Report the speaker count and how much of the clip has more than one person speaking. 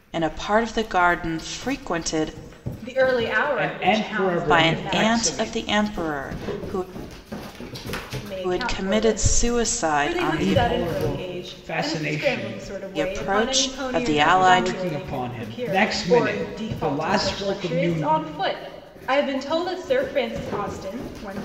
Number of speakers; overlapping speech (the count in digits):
3, about 50%